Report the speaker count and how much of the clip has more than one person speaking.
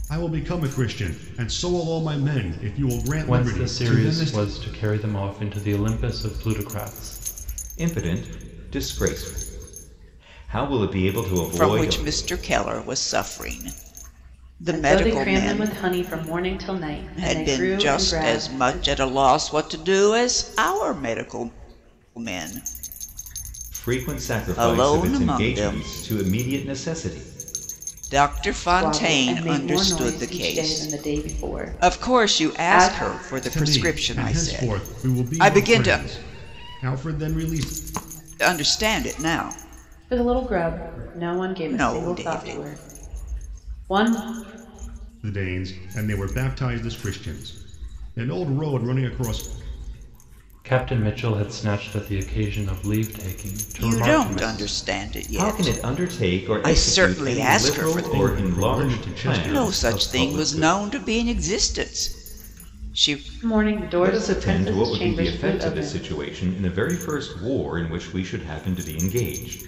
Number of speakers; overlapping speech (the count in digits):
5, about 35%